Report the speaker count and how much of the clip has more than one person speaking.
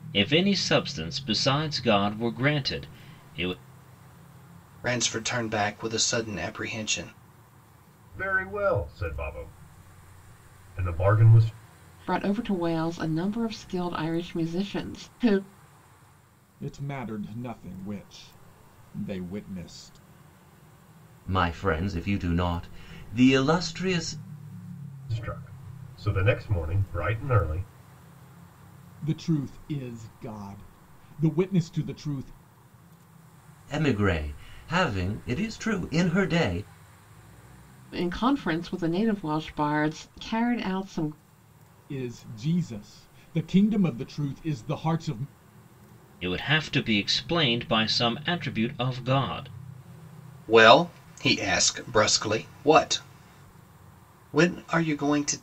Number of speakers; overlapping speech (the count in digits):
6, no overlap